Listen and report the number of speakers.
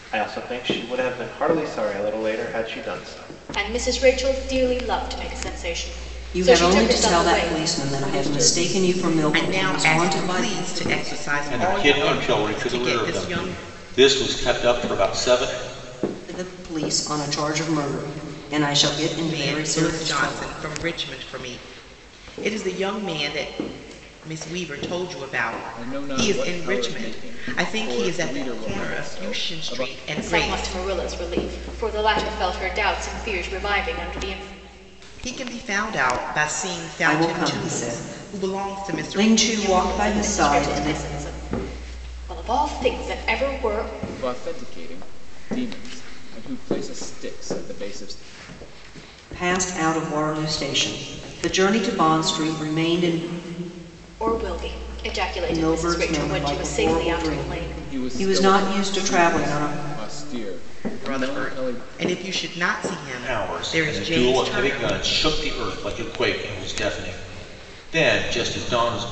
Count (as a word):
six